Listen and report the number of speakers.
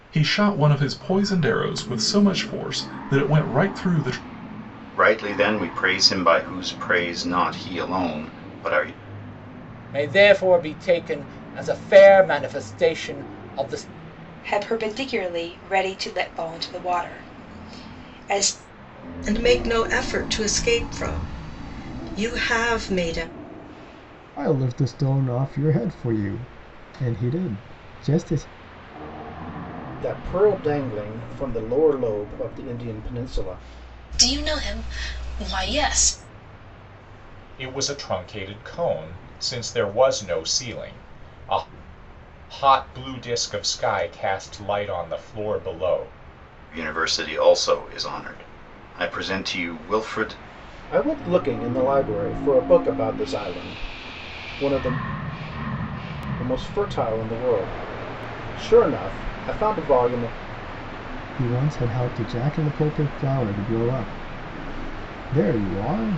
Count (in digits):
9